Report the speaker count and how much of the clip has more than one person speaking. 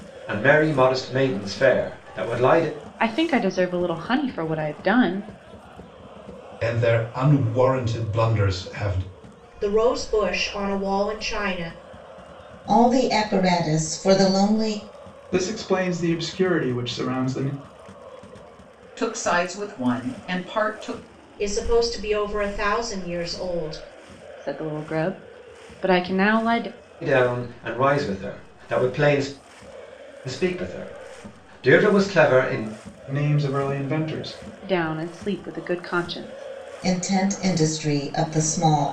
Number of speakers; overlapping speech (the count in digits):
7, no overlap